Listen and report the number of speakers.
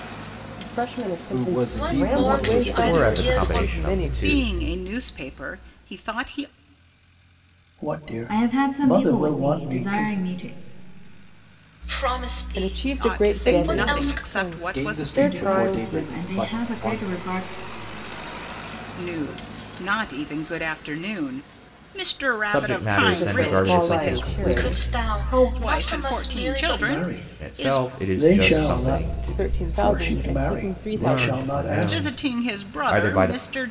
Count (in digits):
9